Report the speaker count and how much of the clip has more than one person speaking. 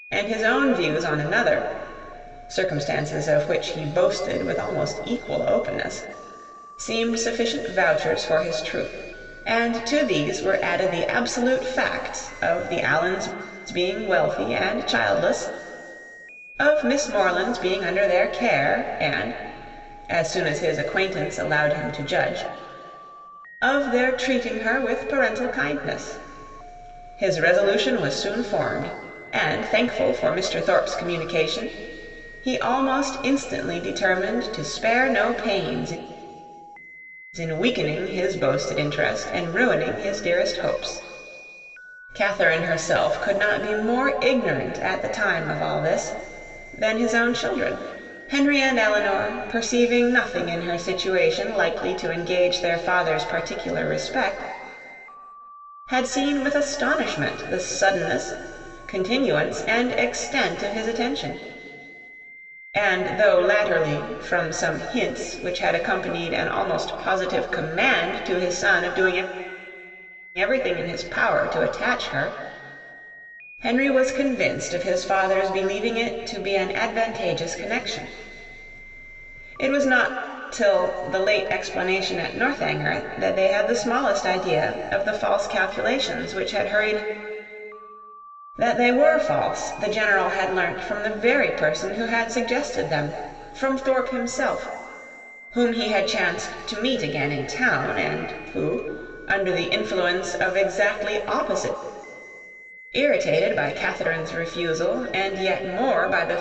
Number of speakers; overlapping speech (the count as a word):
one, no overlap